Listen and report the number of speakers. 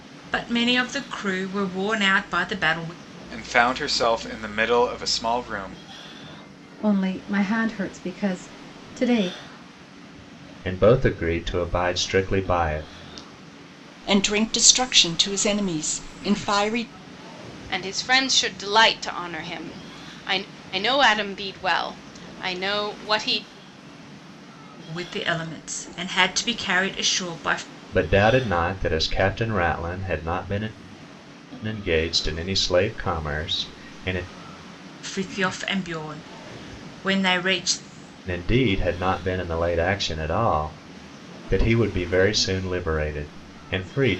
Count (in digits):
6